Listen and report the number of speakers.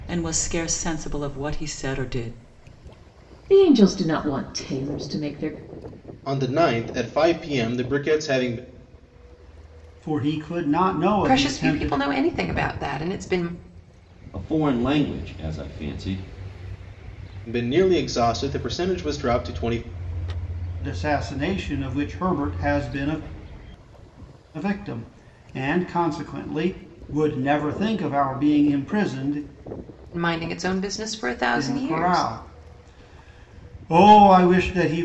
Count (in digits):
6